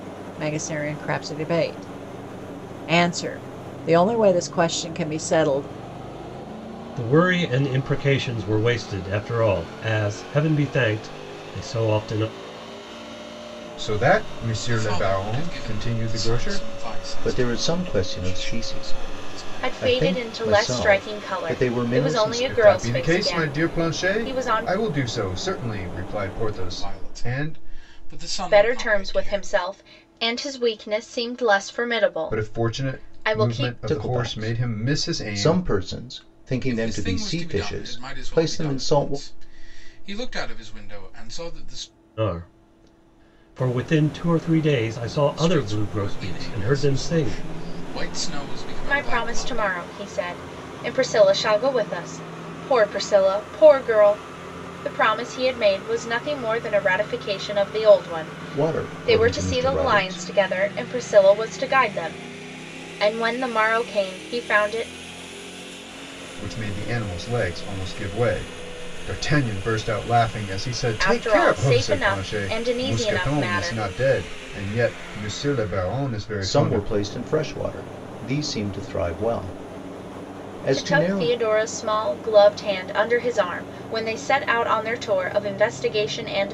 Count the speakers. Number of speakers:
six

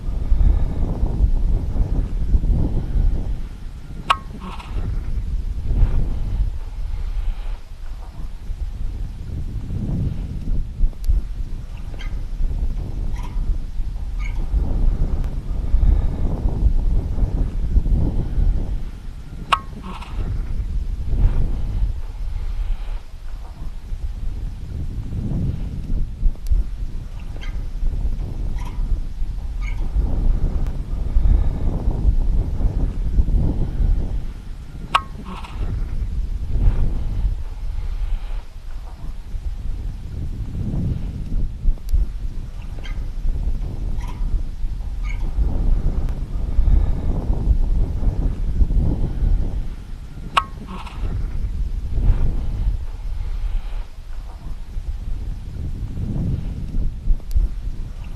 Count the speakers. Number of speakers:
zero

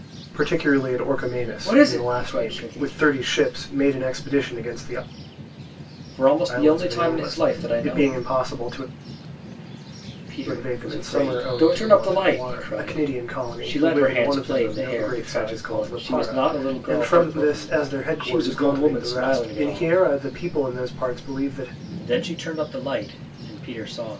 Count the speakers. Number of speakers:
two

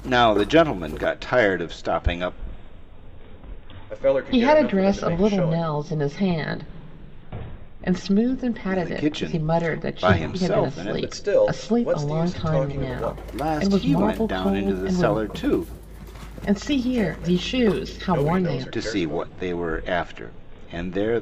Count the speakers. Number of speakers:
three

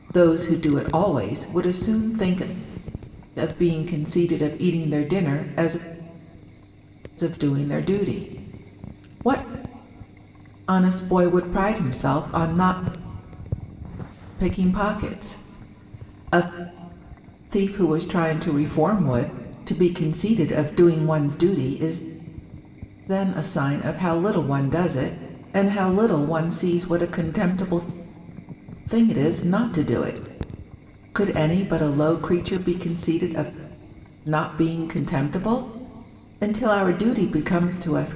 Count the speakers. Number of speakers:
one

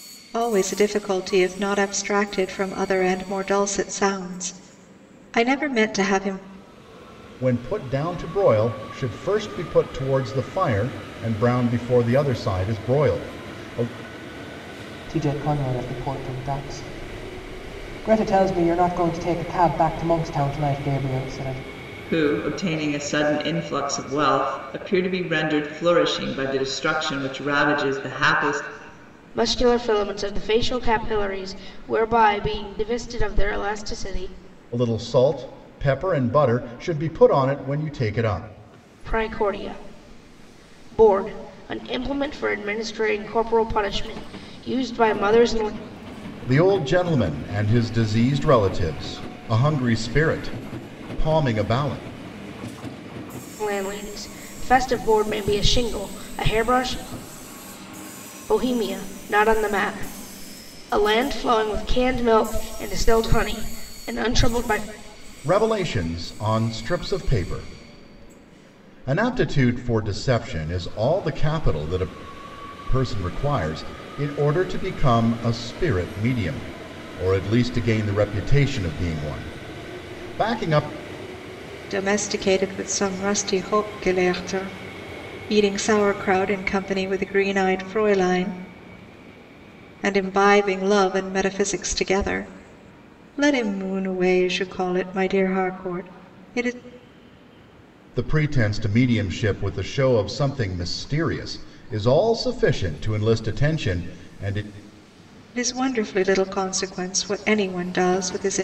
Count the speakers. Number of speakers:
five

